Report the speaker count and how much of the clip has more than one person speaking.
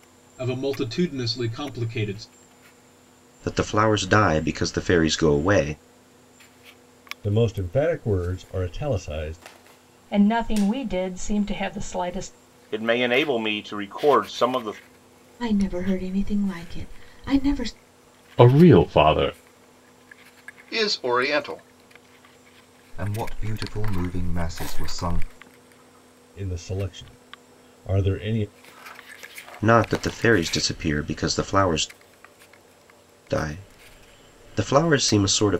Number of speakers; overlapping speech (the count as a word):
nine, no overlap